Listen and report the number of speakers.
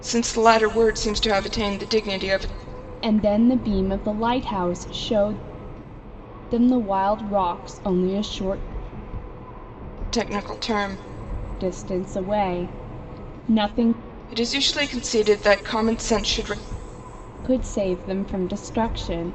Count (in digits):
2